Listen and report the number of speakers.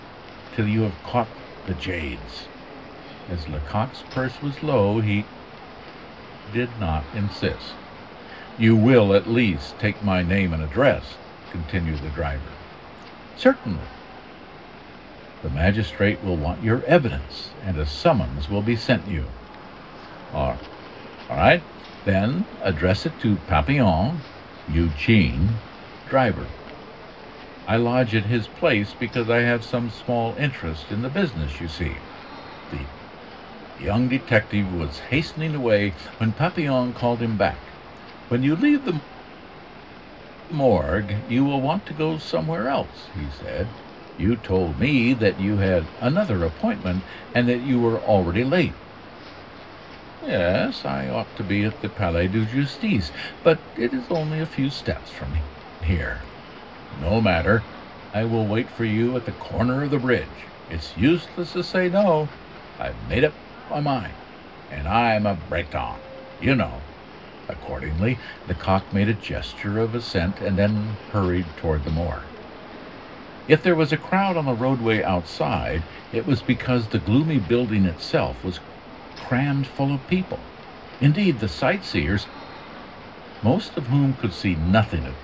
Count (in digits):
1